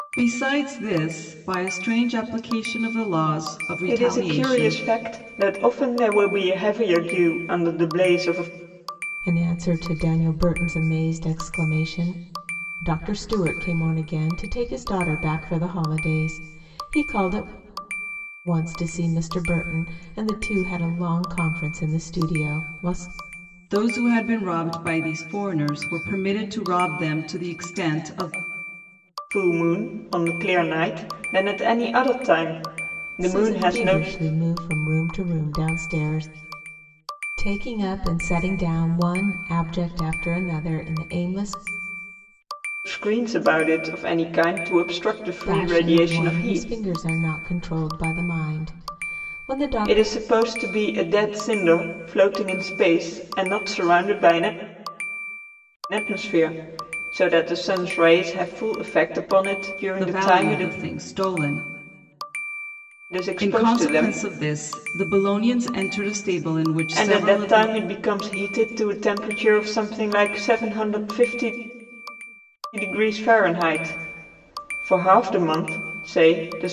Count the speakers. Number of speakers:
3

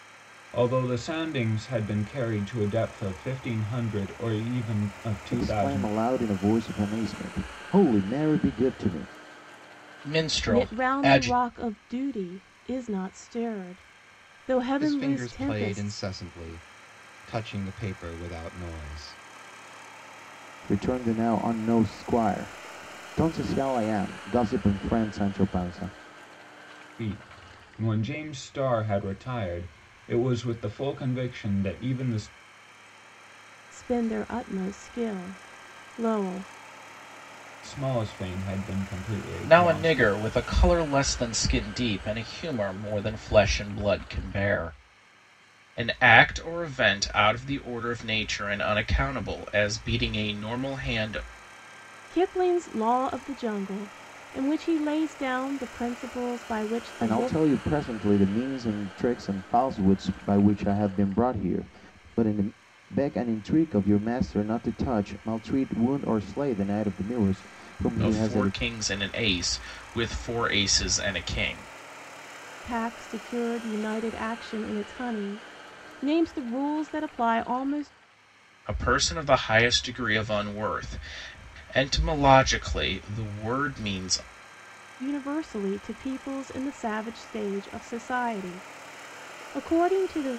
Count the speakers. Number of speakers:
5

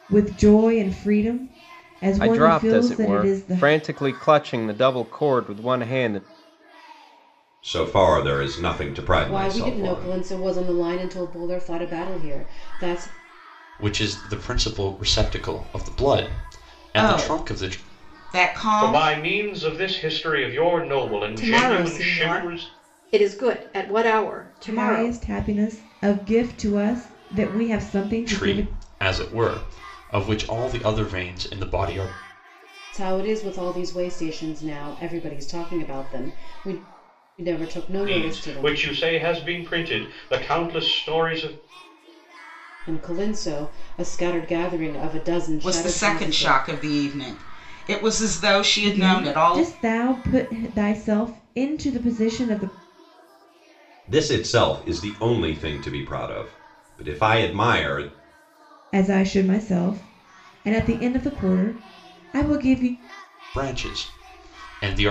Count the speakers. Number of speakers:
8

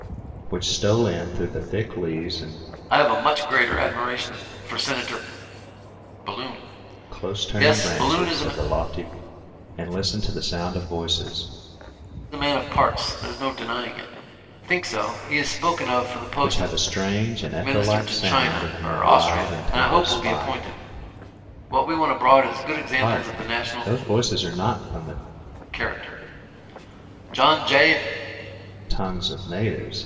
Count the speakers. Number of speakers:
2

